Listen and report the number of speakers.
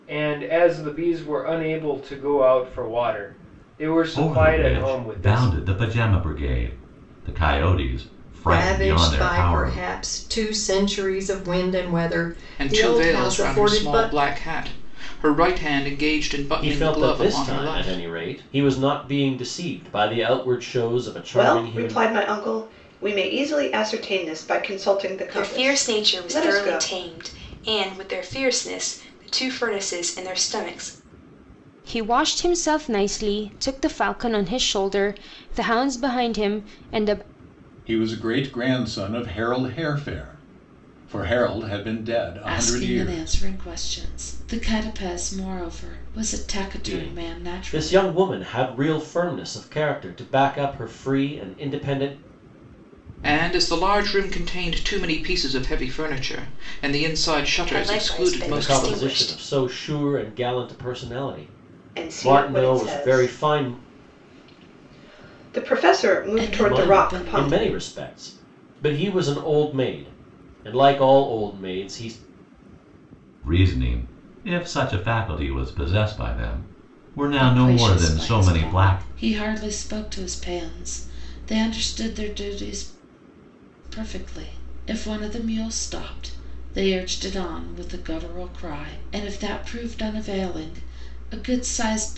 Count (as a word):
ten